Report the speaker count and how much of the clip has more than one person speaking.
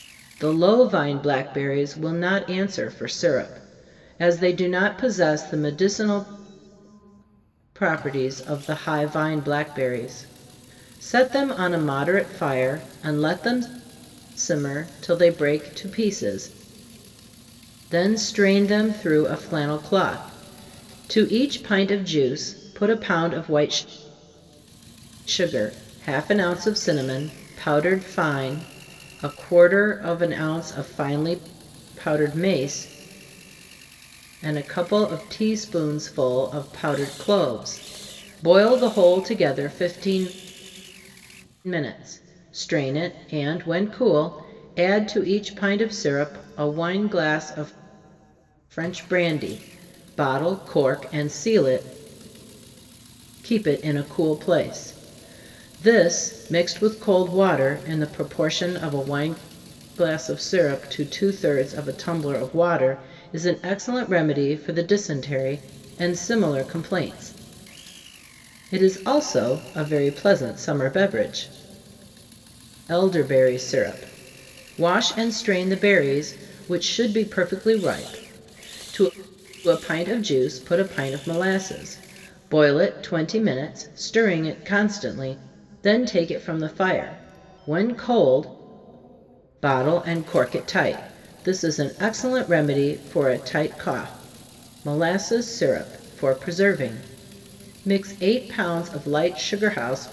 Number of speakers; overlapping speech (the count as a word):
one, no overlap